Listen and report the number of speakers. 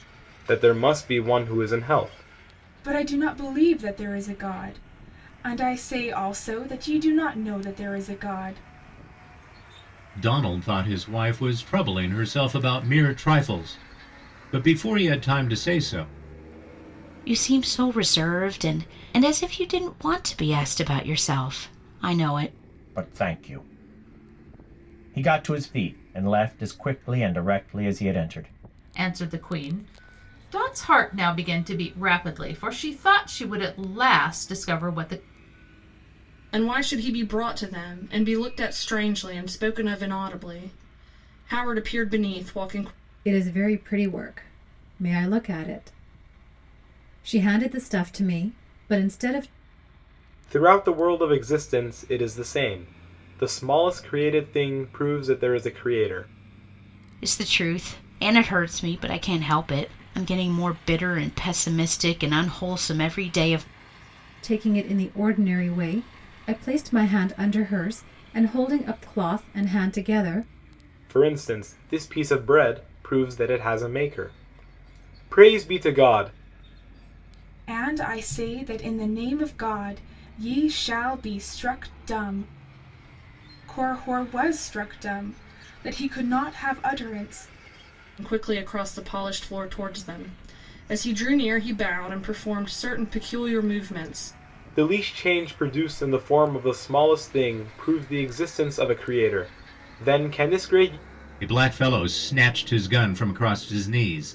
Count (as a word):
eight